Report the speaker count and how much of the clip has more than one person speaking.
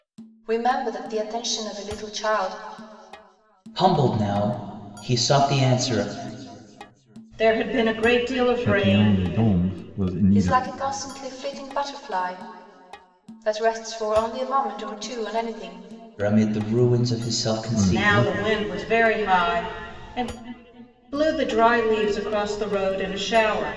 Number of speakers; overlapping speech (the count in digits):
4, about 10%